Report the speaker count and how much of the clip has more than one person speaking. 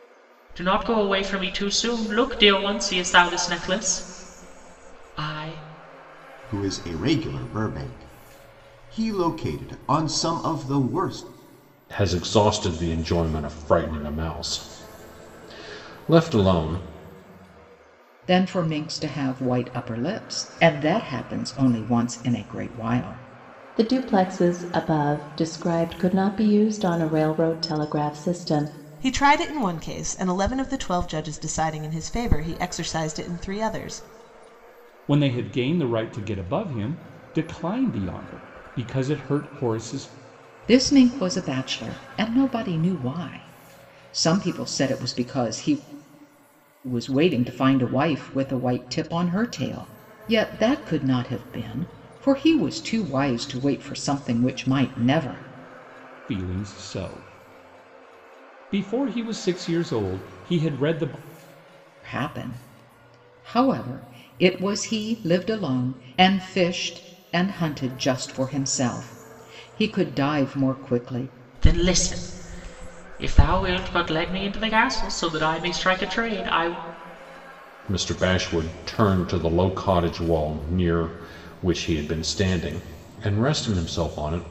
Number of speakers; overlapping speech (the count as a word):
seven, no overlap